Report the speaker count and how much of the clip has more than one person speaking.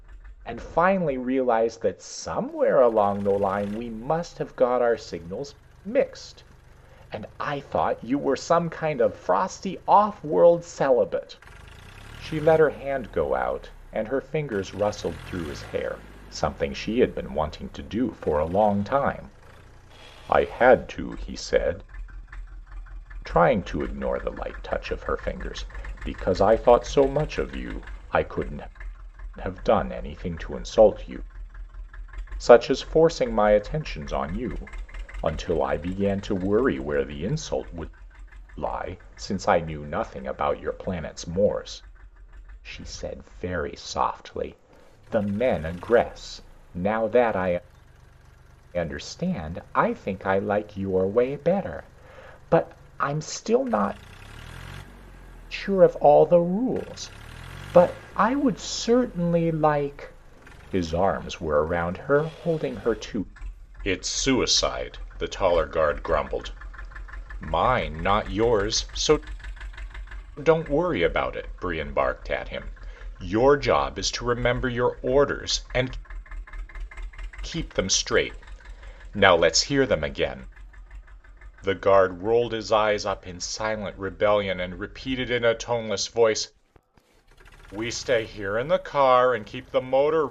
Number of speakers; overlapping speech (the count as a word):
one, no overlap